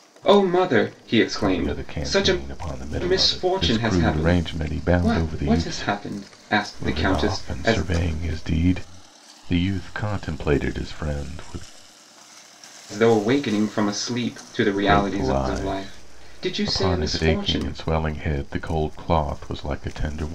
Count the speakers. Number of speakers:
two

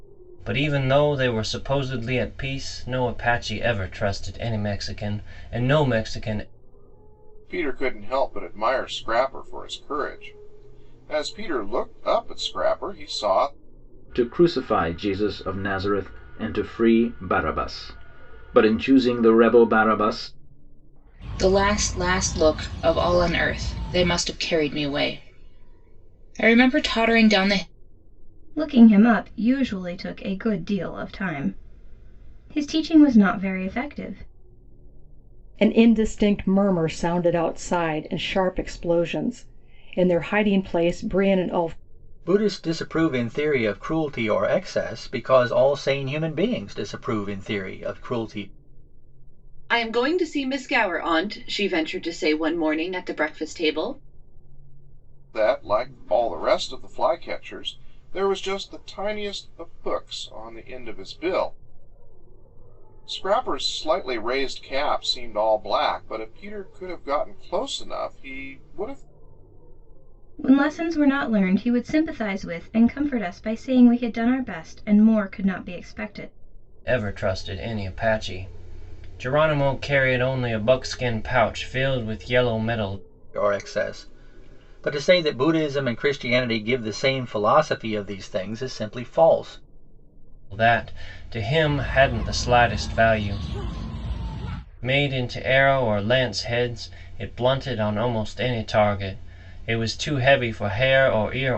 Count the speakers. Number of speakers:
eight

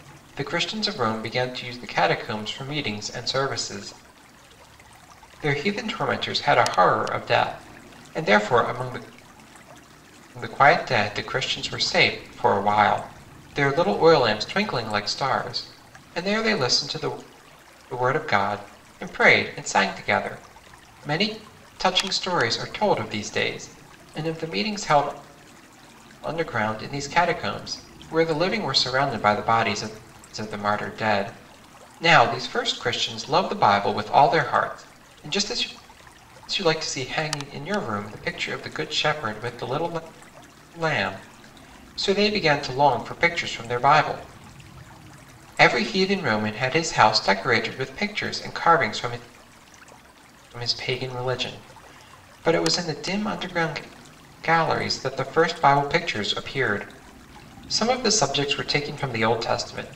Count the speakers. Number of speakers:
one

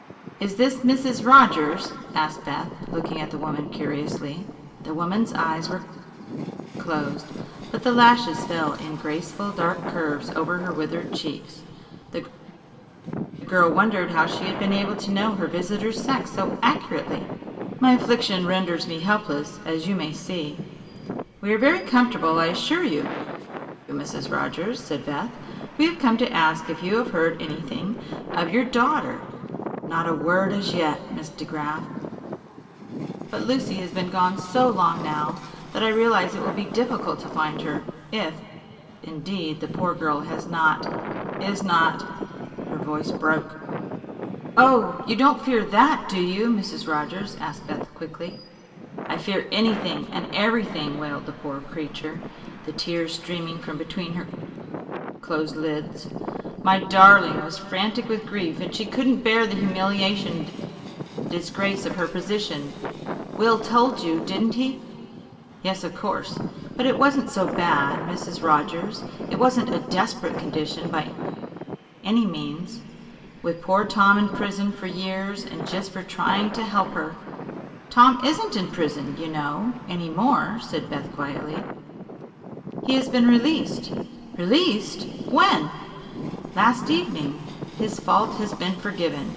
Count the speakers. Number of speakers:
one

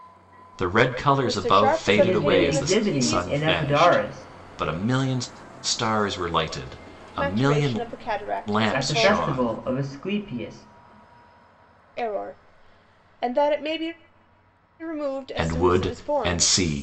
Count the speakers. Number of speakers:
three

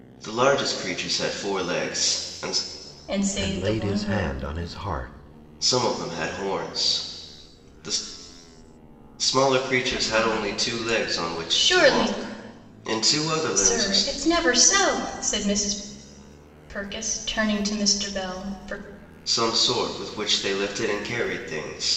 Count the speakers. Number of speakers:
three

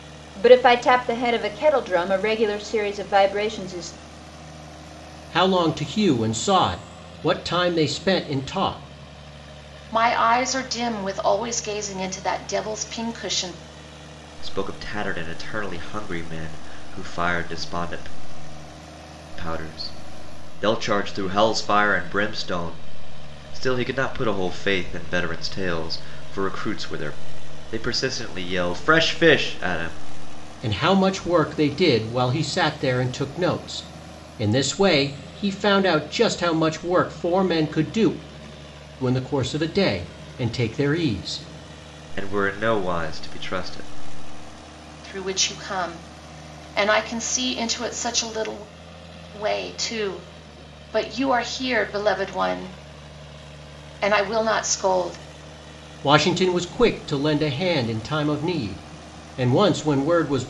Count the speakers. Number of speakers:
four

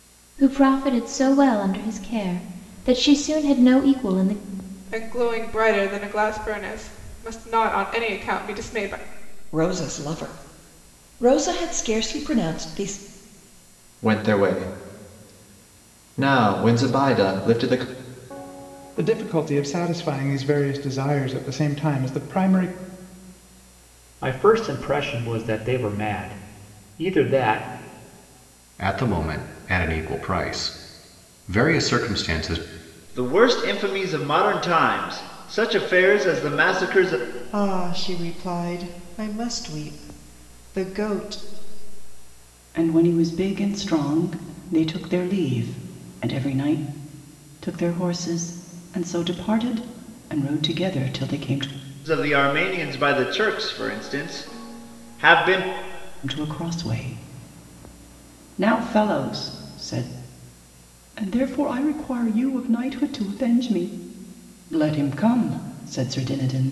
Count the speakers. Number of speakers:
ten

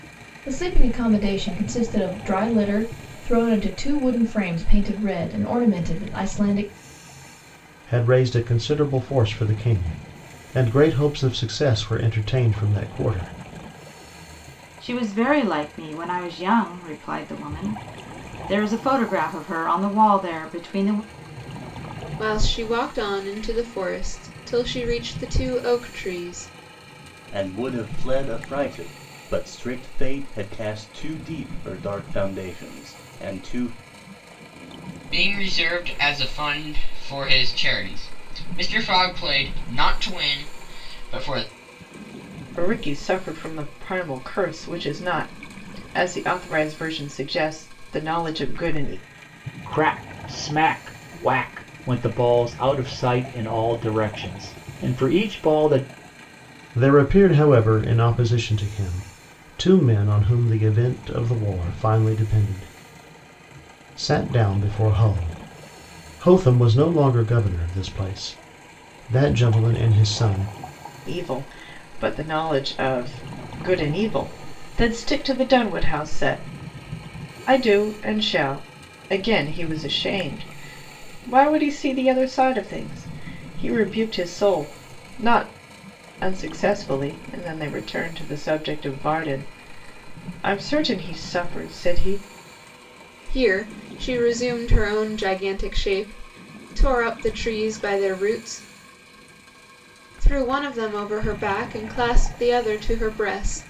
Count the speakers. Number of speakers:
eight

